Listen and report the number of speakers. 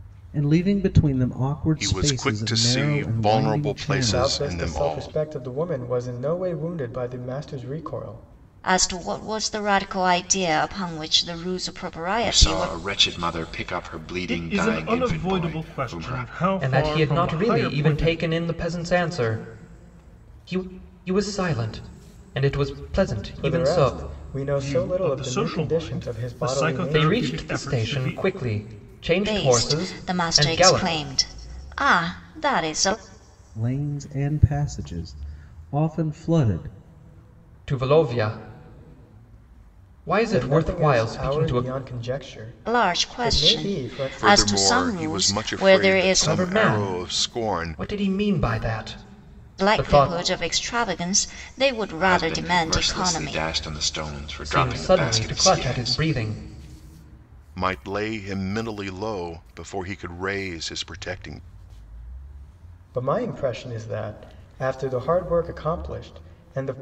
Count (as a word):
seven